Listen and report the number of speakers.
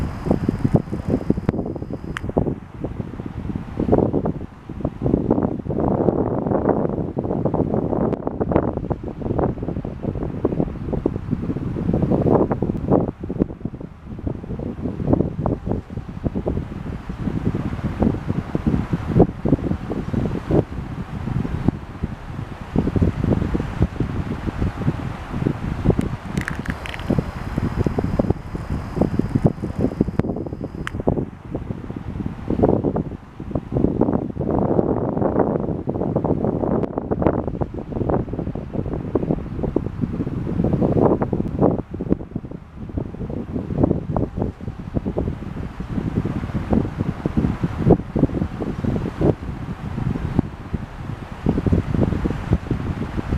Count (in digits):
0